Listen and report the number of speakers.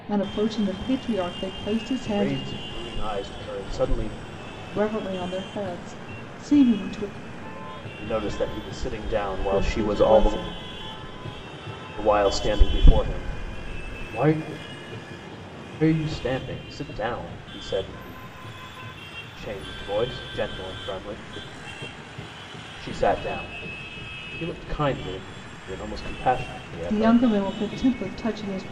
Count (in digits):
2